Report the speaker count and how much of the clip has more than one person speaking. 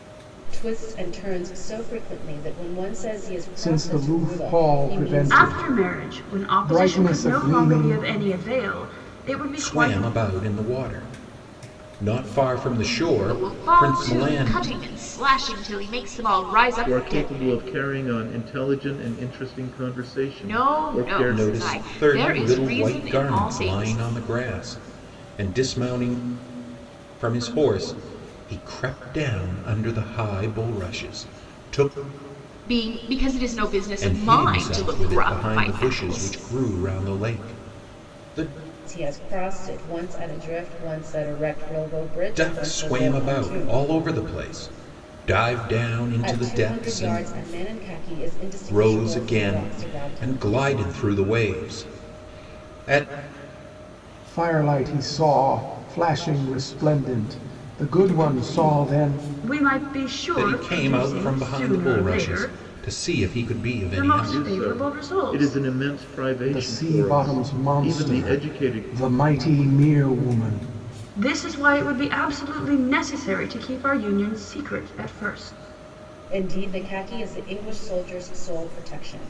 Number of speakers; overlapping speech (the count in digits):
6, about 32%